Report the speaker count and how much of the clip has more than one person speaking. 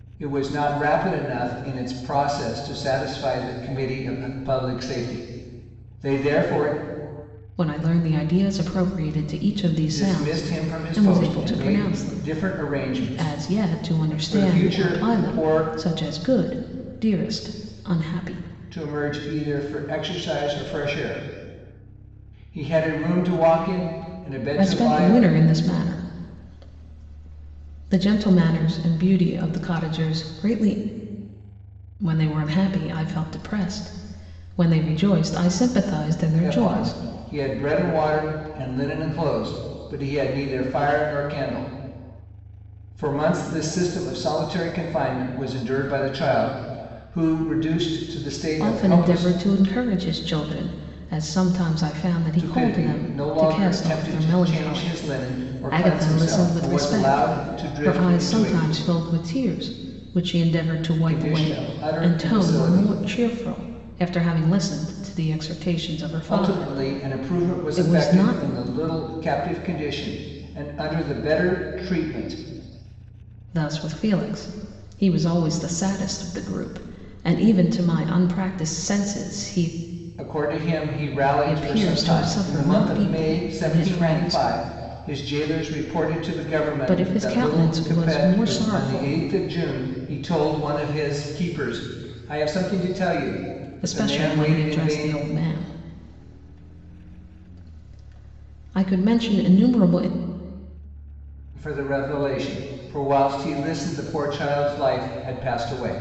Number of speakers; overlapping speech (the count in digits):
2, about 22%